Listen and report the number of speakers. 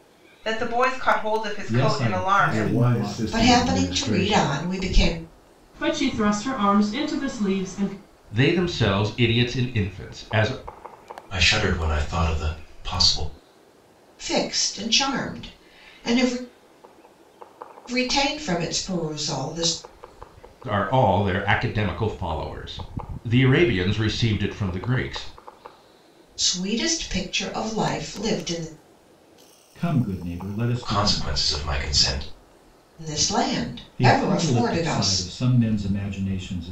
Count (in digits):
7